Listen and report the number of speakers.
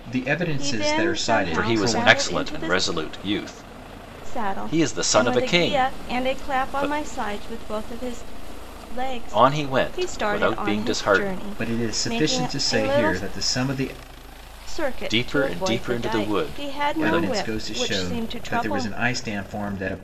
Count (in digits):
3